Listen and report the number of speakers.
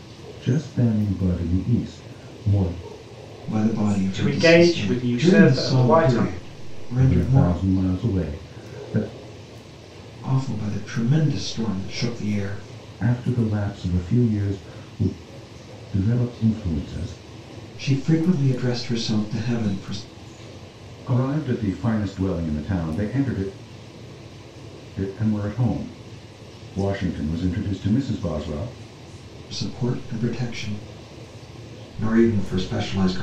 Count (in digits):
3